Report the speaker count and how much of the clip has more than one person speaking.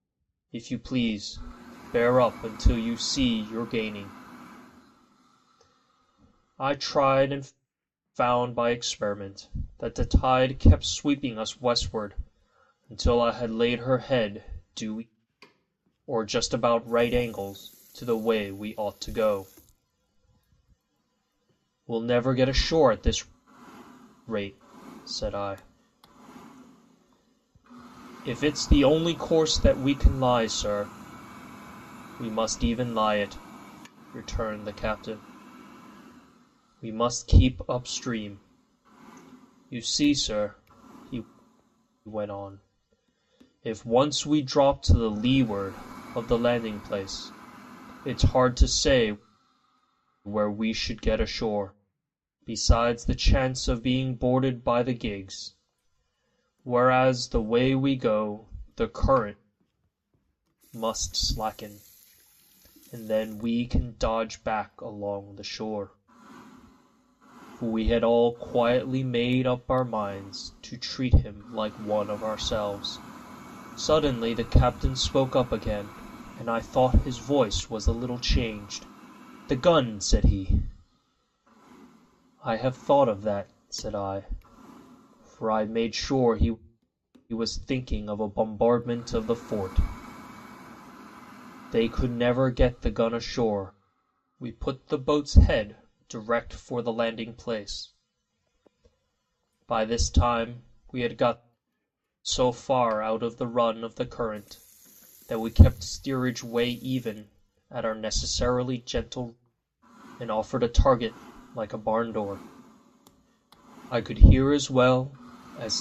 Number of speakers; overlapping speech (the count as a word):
one, no overlap